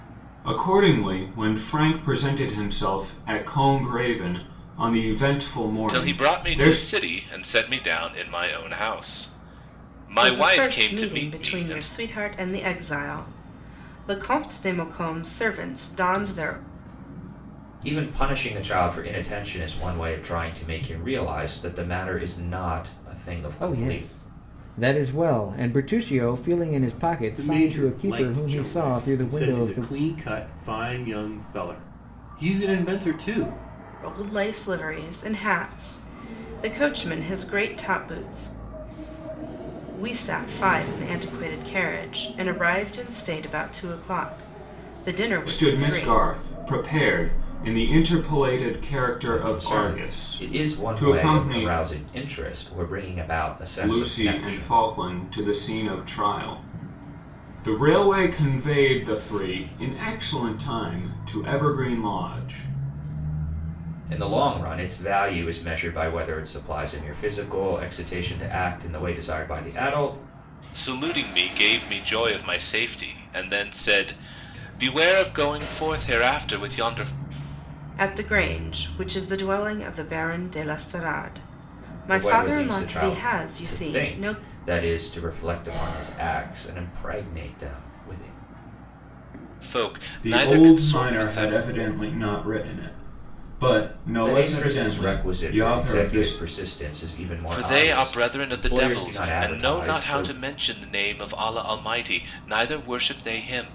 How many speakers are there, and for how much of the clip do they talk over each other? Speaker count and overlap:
6, about 18%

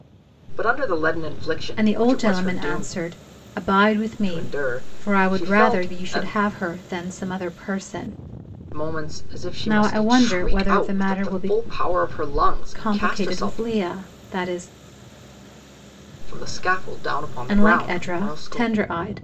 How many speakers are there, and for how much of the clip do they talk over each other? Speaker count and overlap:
2, about 39%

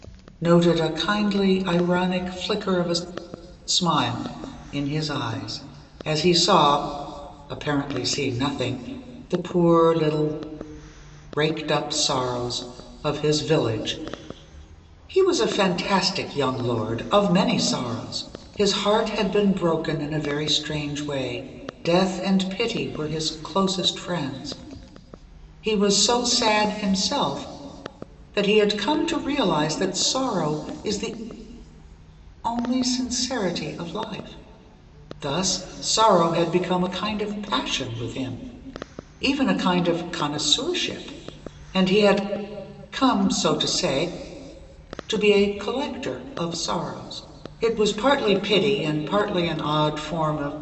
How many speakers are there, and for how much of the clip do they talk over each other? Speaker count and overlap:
1, no overlap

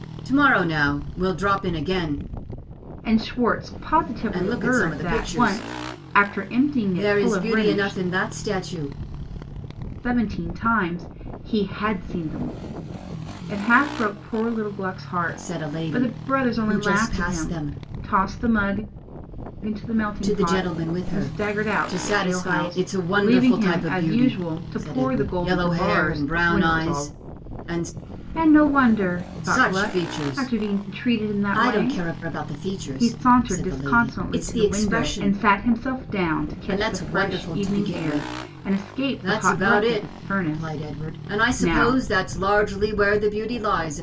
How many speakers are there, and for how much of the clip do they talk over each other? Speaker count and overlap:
2, about 50%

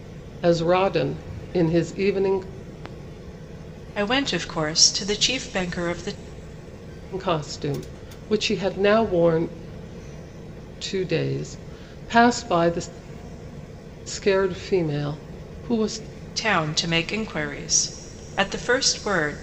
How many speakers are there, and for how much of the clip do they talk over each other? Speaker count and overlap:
2, no overlap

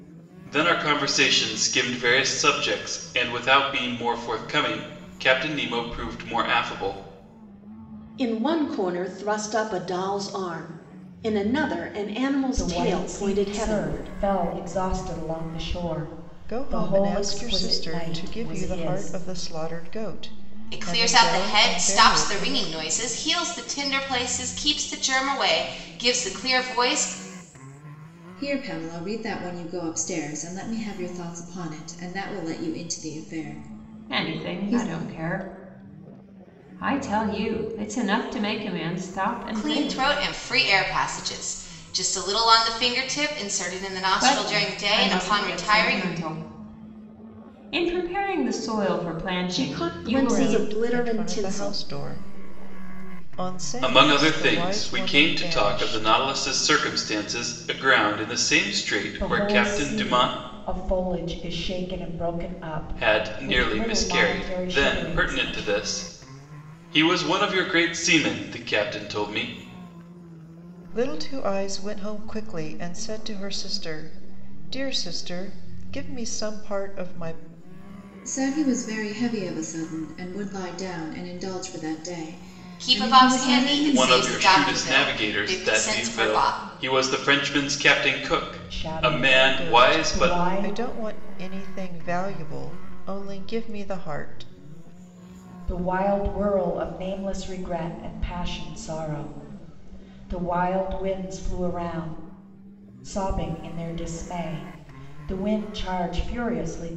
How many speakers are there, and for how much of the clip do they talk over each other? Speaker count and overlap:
7, about 23%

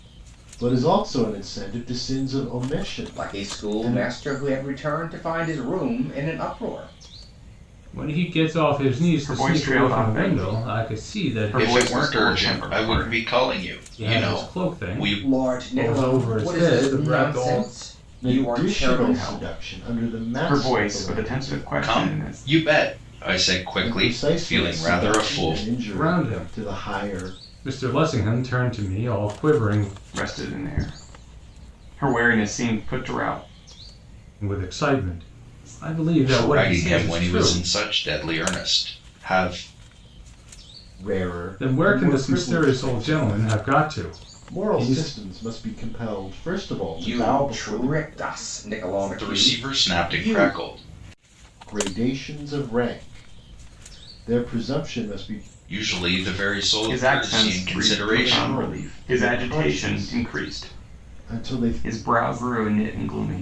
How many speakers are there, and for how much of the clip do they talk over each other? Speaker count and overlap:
5, about 43%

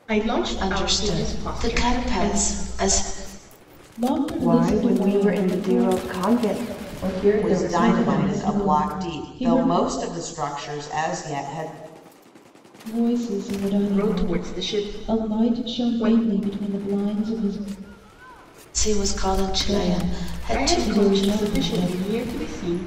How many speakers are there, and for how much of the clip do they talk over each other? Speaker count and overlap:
6, about 47%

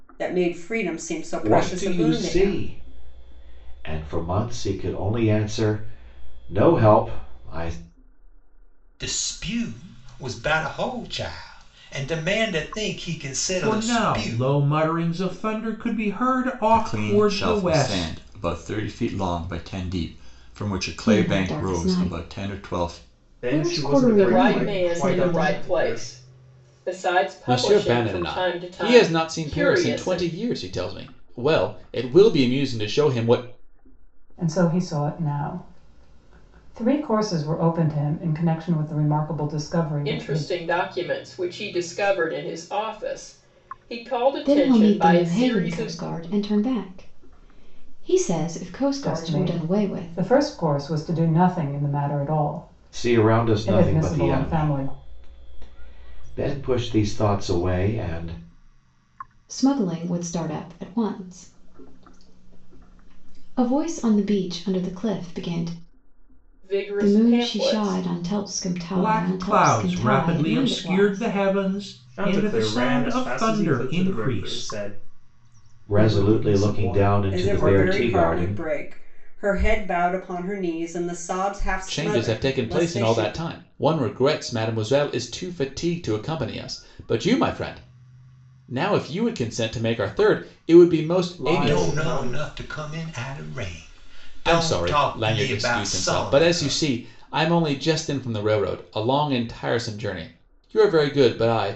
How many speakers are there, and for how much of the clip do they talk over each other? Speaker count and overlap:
10, about 30%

